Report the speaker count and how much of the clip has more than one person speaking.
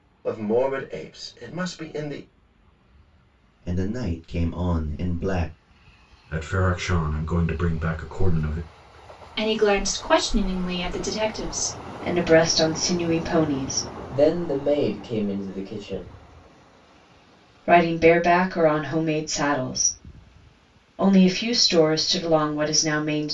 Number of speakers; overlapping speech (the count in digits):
6, no overlap